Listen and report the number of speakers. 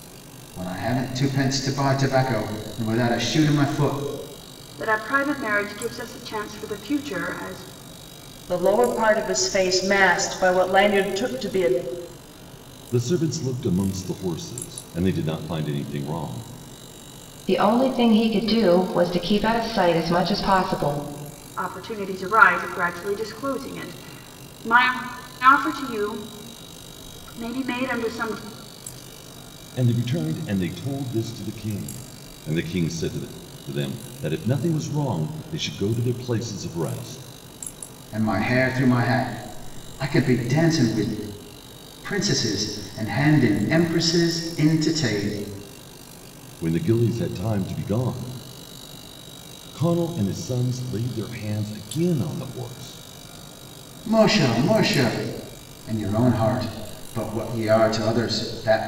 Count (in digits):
5